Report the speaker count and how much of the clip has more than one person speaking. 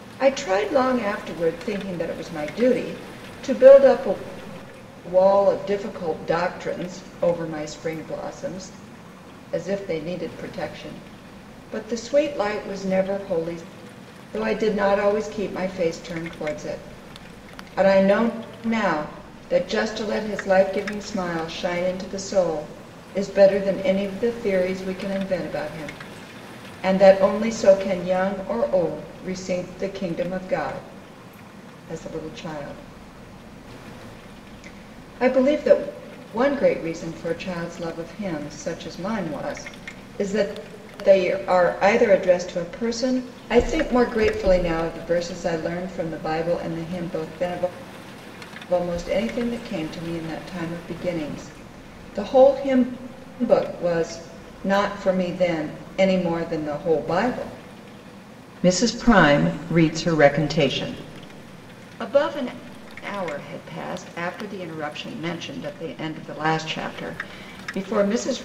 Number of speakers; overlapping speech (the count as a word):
one, no overlap